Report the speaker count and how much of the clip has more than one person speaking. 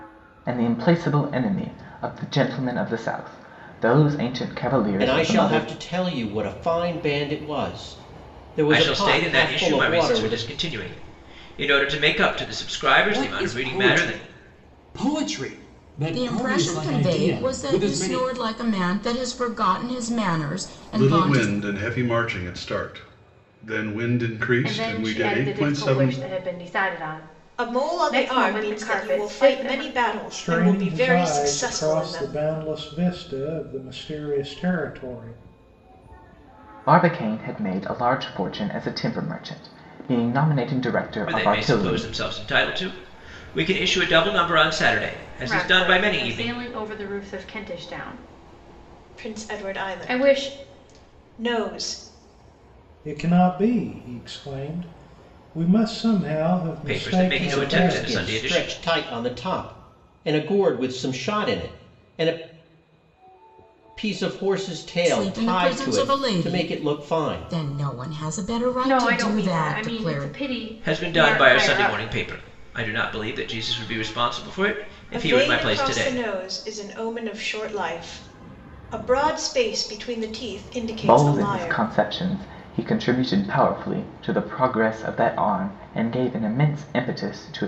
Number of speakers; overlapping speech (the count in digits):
9, about 28%